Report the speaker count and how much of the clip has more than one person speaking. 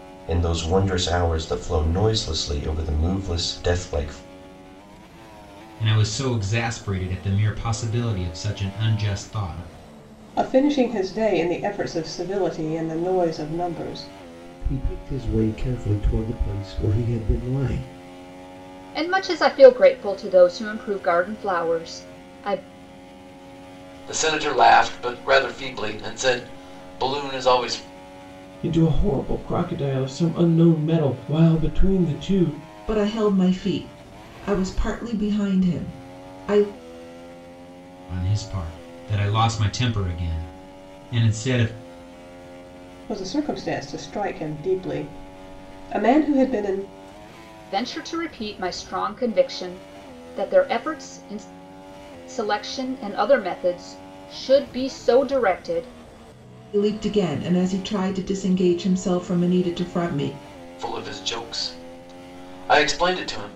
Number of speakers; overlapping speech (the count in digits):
8, no overlap